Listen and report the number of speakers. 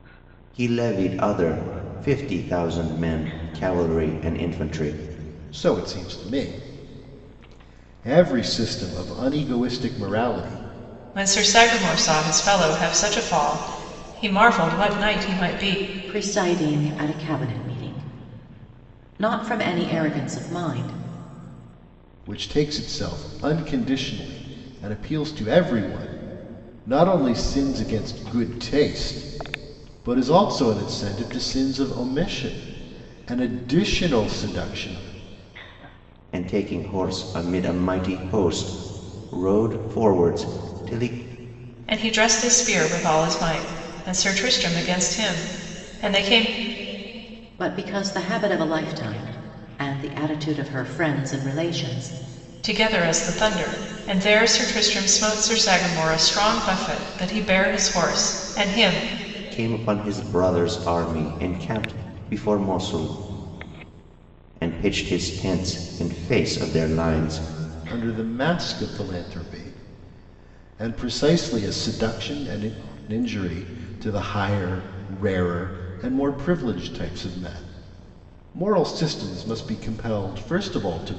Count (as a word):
four